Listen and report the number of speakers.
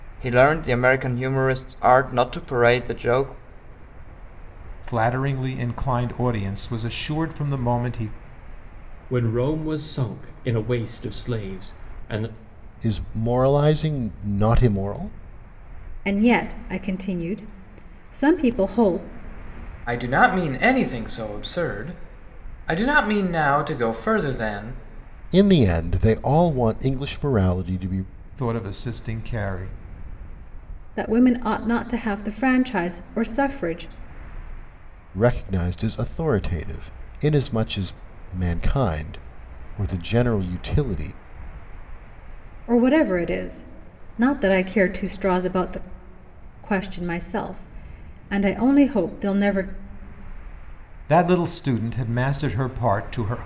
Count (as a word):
six